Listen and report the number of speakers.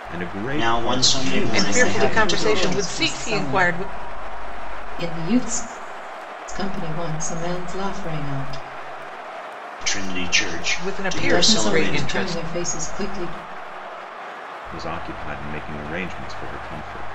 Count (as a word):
four